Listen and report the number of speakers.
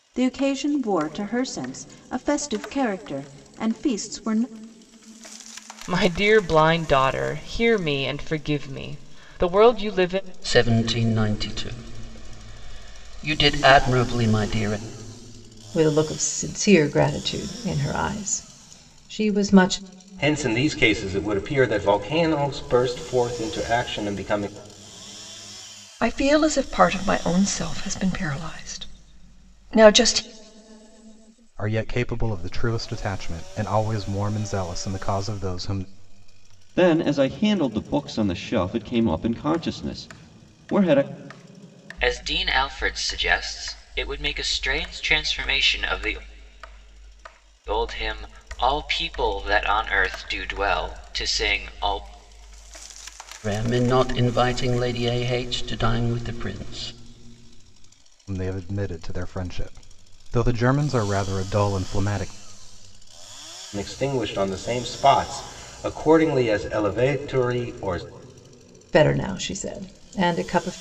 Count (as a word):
nine